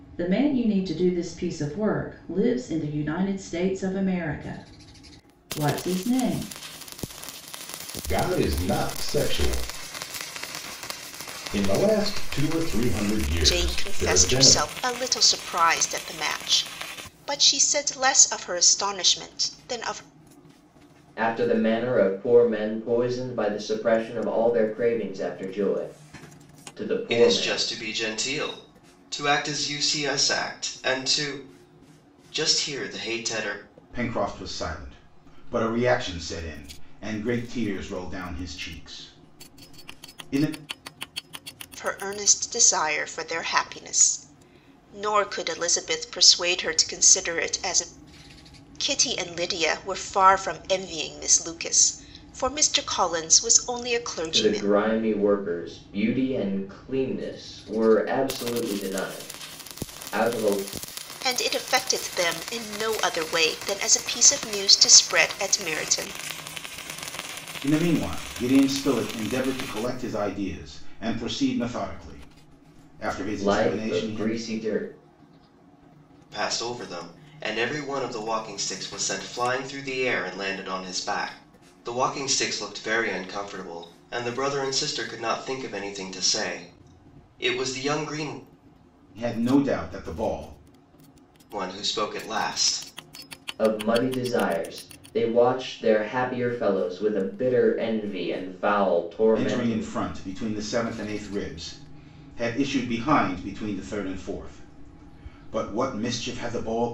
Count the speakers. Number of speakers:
6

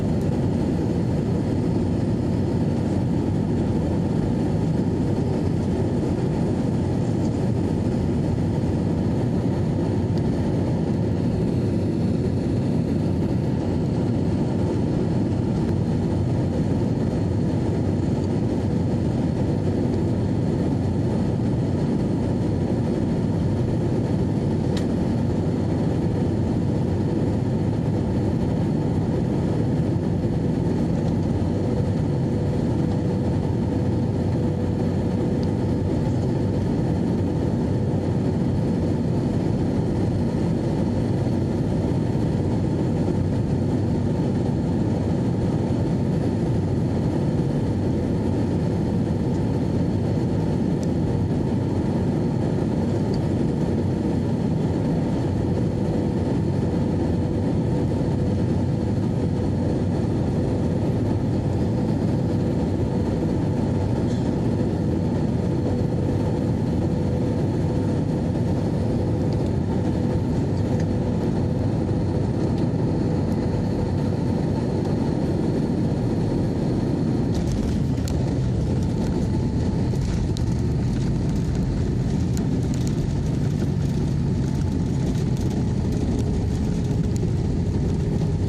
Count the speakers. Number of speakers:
0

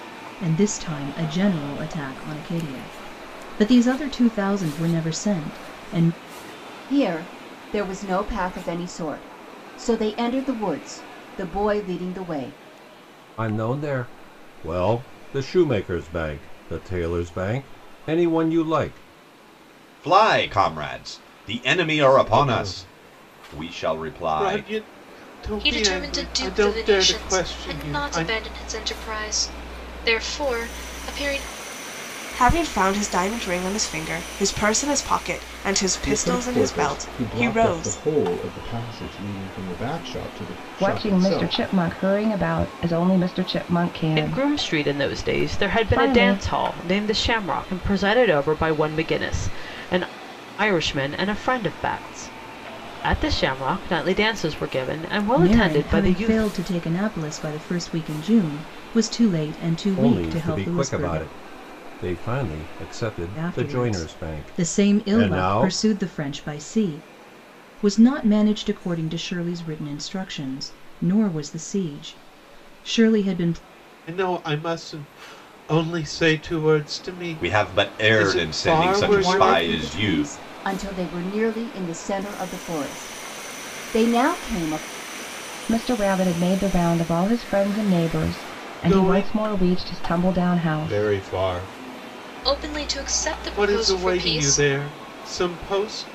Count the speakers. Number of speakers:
10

